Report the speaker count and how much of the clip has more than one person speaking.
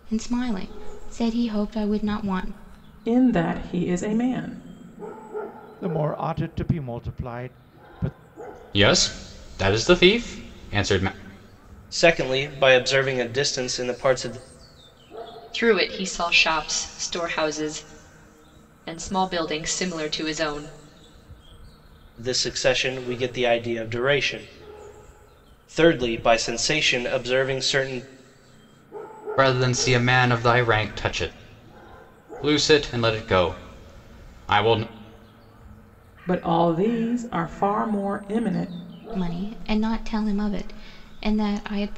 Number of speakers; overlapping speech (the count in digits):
6, no overlap